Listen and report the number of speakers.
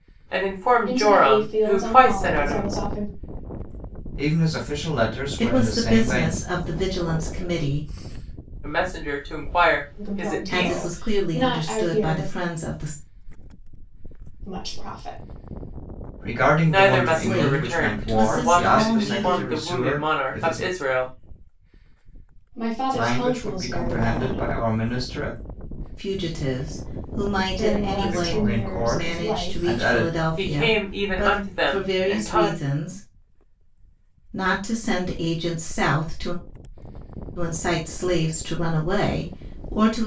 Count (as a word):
four